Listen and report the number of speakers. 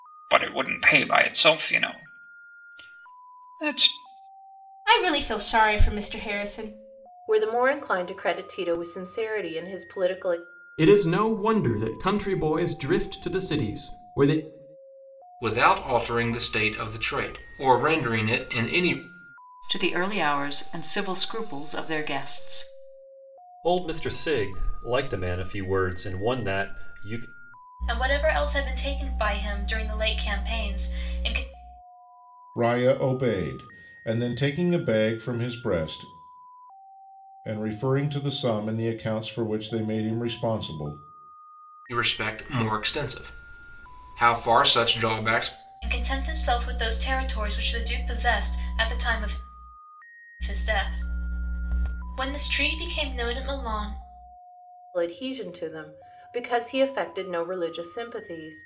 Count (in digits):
9